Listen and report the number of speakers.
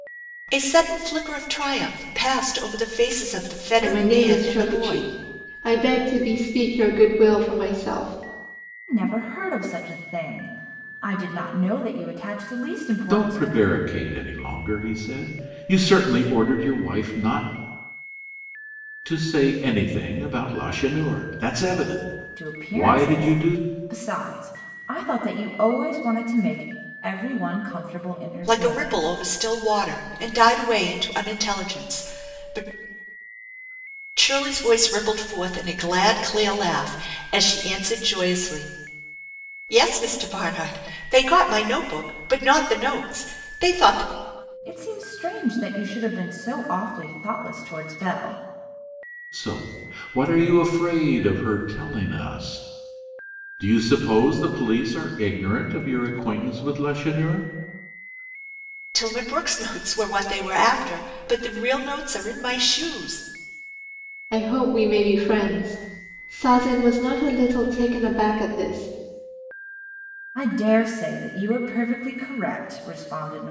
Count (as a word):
four